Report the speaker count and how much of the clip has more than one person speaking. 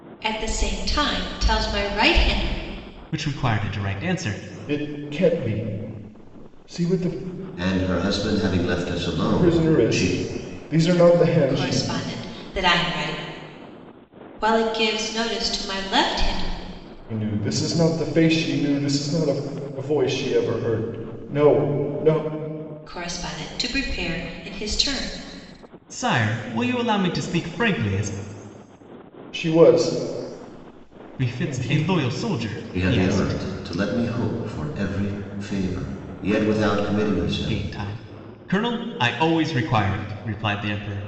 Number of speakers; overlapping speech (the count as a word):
four, about 7%